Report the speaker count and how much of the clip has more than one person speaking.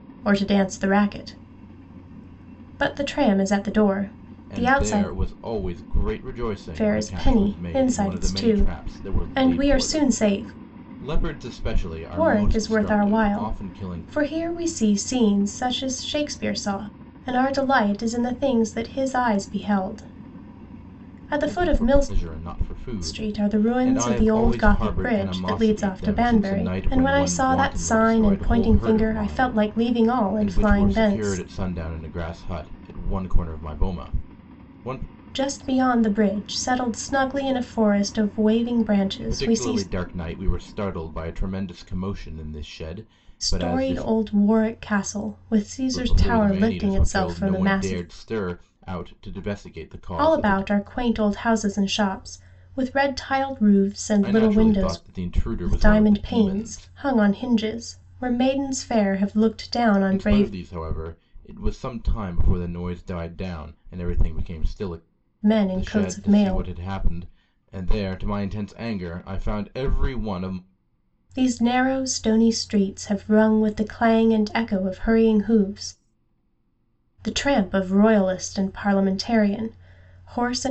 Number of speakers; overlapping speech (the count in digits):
2, about 28%